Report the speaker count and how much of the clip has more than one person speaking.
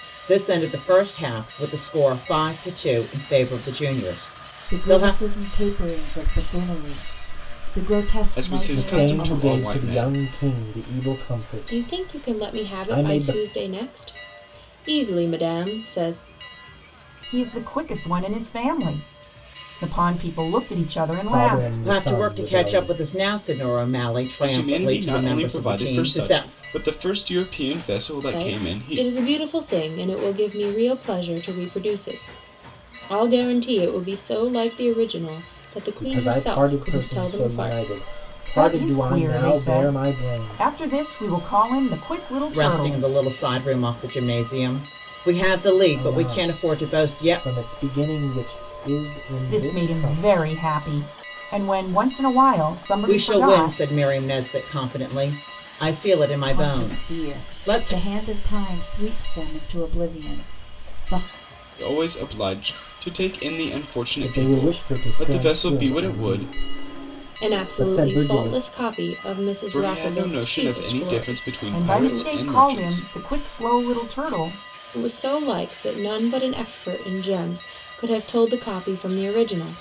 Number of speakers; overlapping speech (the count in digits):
6, about 32%